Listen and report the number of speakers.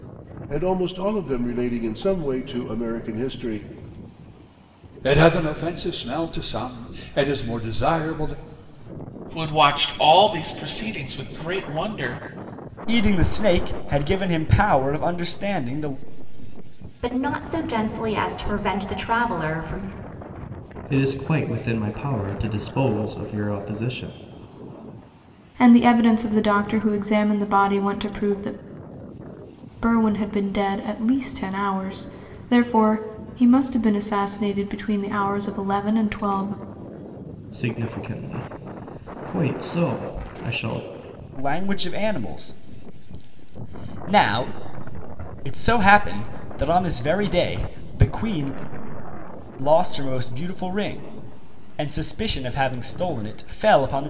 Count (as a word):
seven